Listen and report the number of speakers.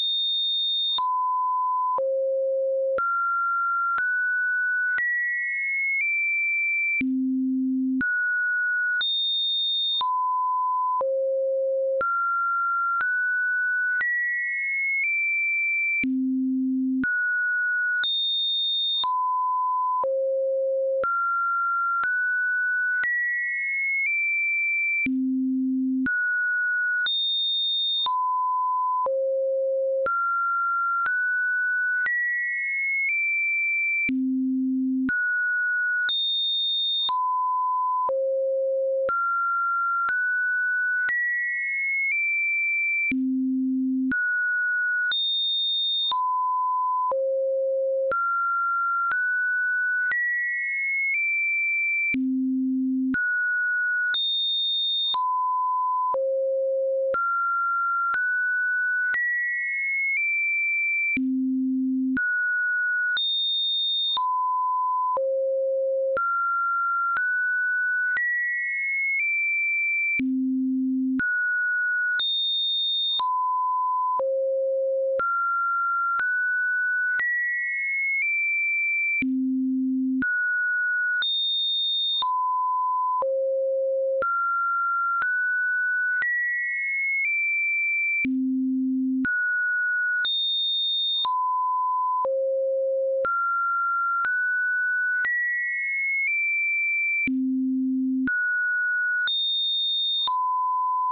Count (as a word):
zero